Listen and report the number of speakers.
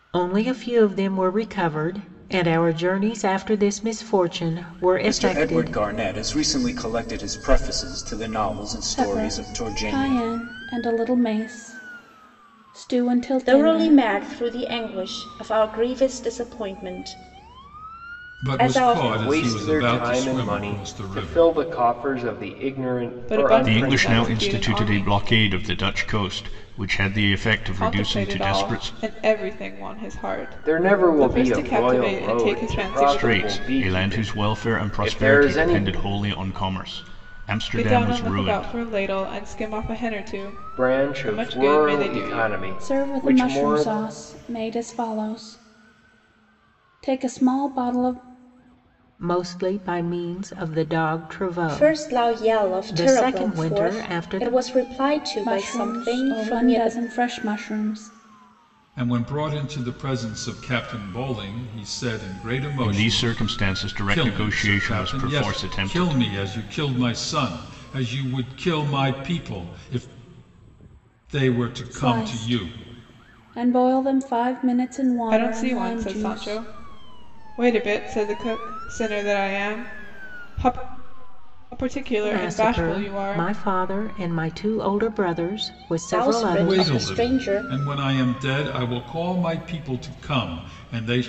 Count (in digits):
8